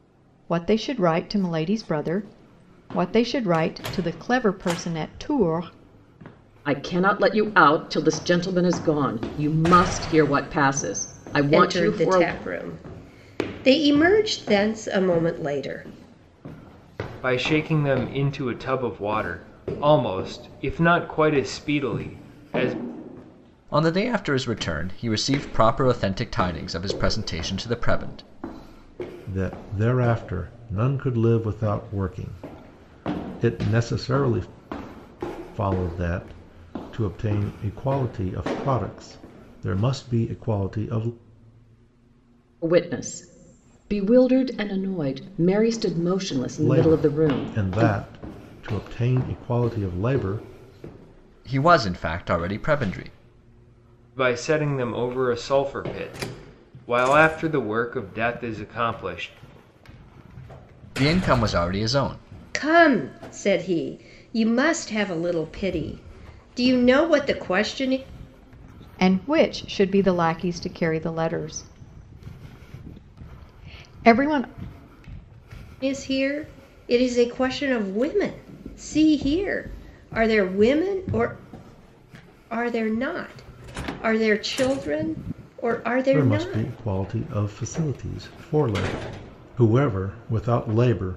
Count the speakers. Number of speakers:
6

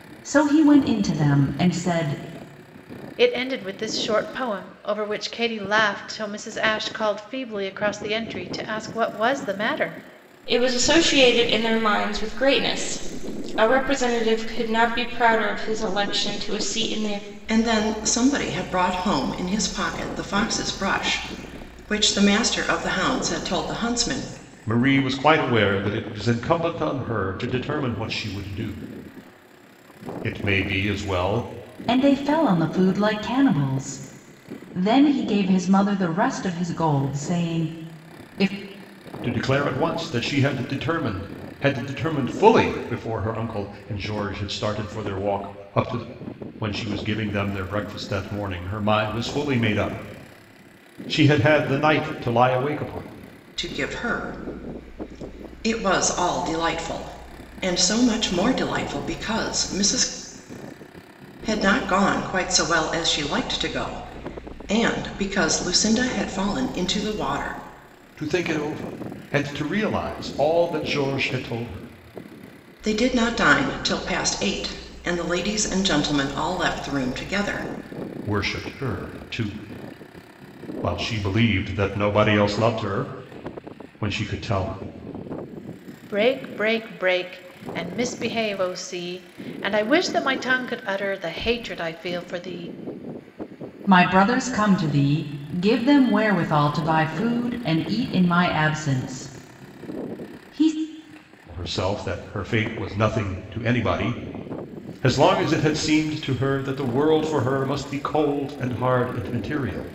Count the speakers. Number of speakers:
5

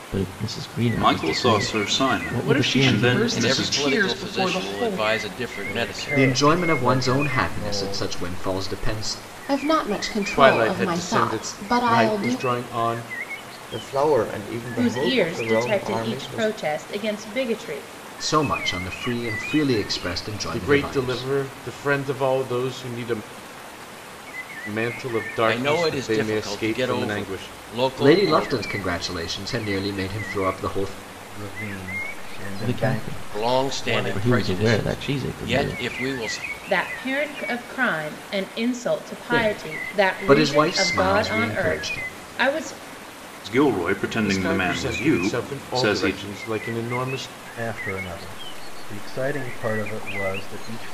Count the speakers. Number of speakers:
10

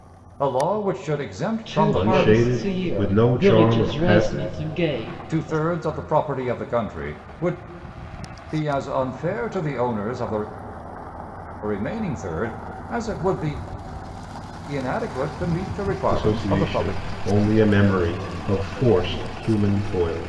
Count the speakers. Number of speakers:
3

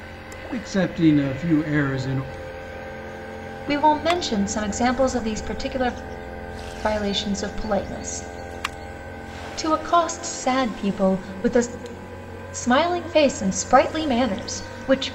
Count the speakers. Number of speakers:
2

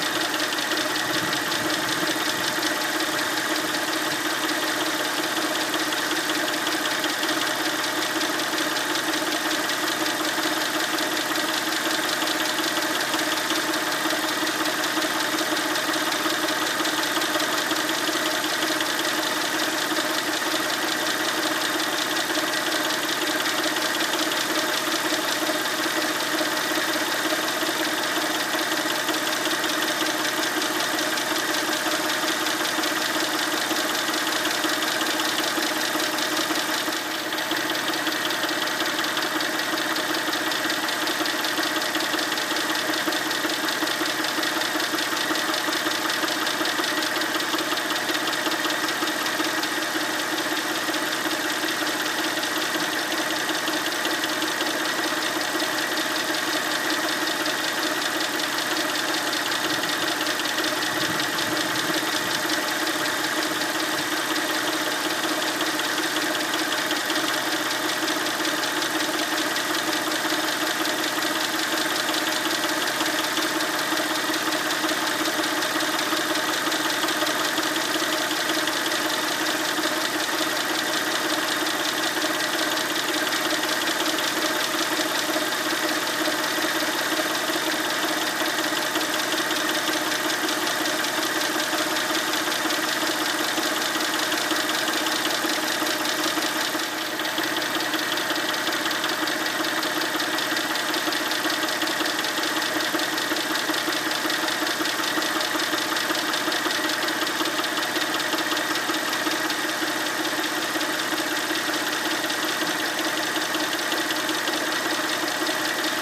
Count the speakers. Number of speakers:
0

